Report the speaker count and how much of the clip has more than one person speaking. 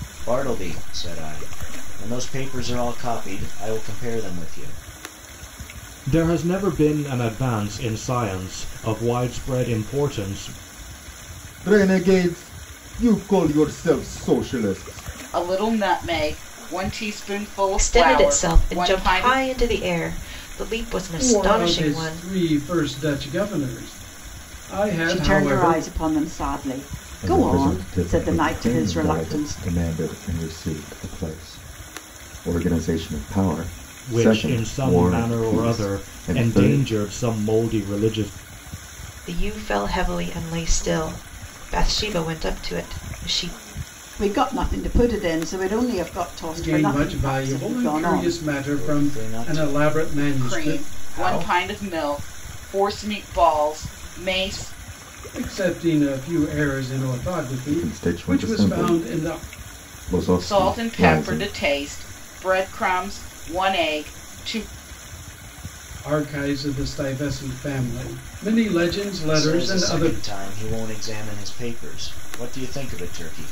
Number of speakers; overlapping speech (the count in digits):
7, about 24%